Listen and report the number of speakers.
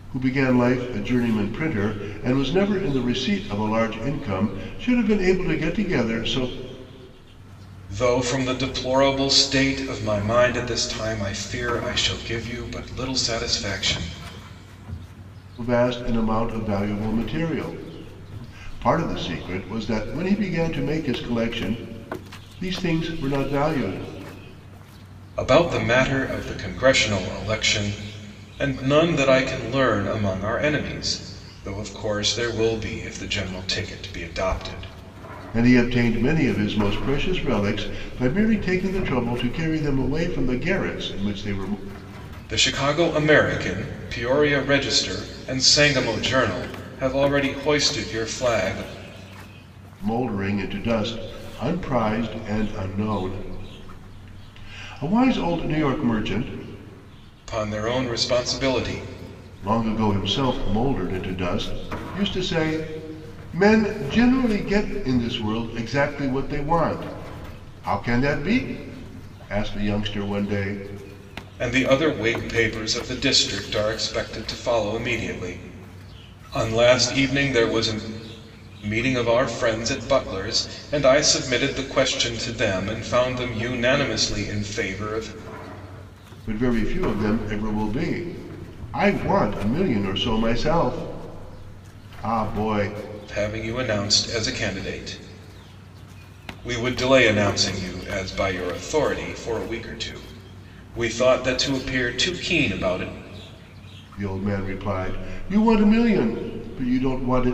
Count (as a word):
two